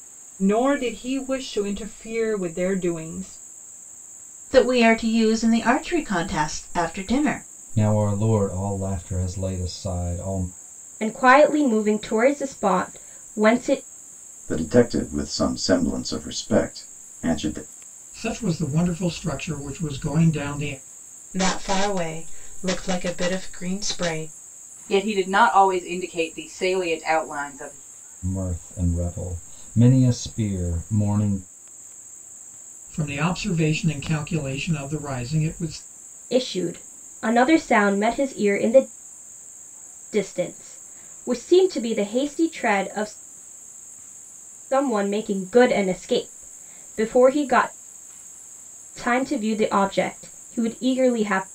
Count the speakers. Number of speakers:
eight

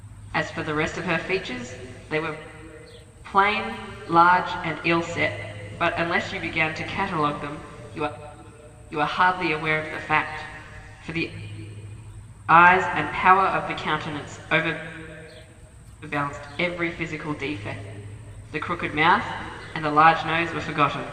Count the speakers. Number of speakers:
one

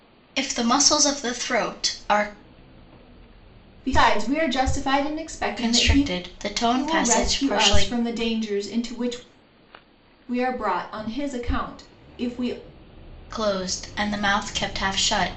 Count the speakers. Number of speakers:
two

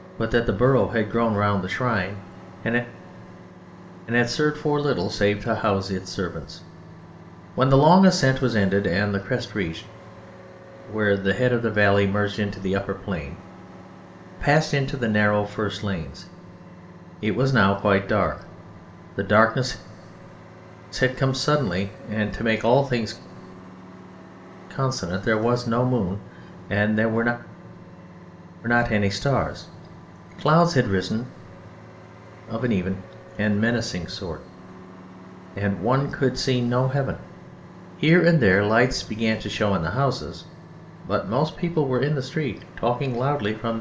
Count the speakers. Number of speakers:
one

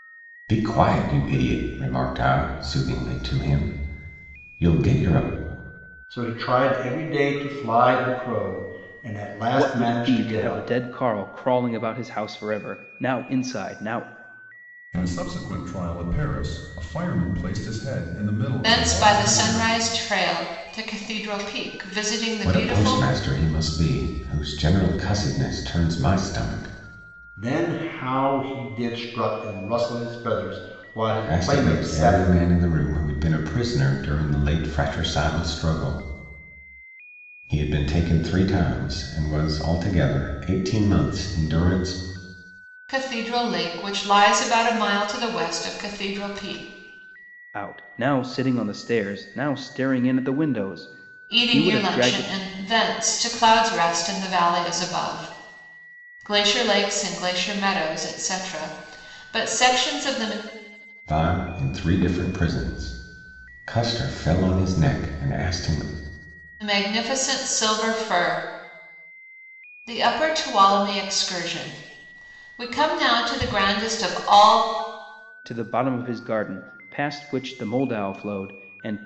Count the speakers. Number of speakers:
five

